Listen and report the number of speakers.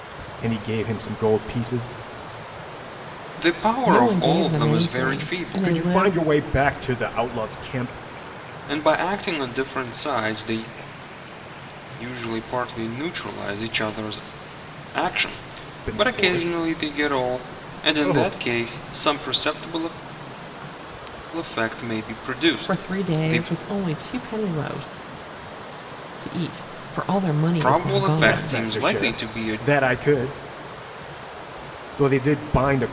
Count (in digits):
3